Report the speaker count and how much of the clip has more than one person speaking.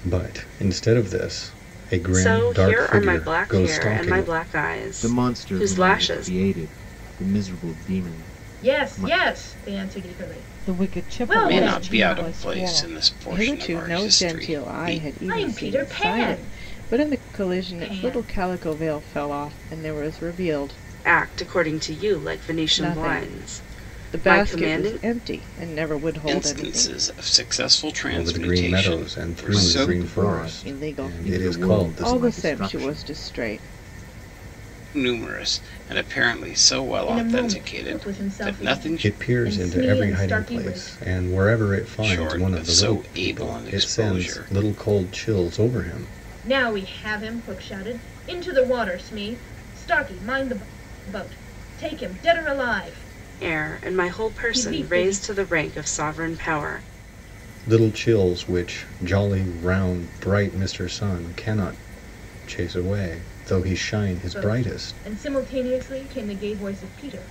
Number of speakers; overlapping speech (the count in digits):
7, about 42%